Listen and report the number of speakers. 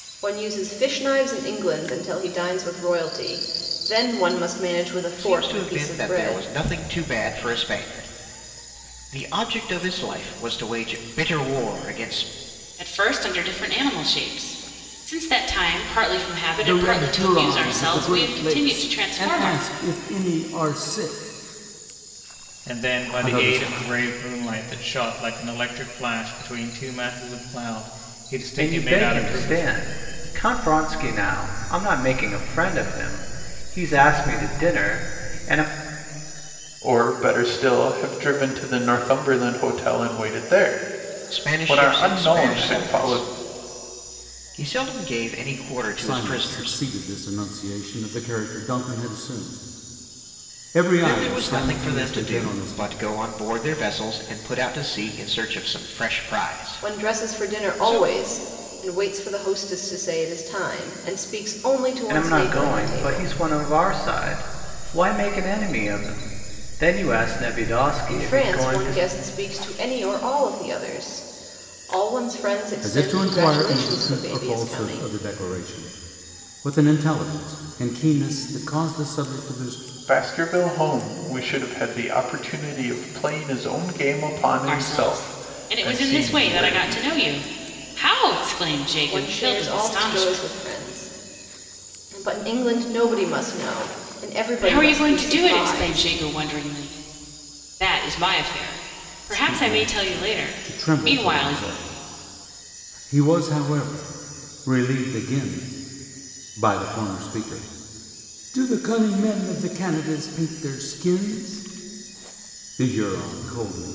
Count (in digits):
7